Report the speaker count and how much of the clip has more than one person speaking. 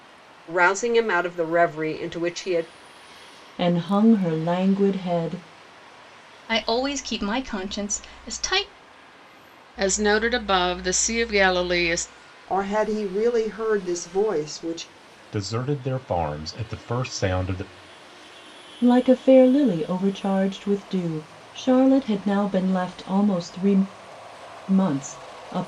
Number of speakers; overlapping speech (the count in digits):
6, no overlap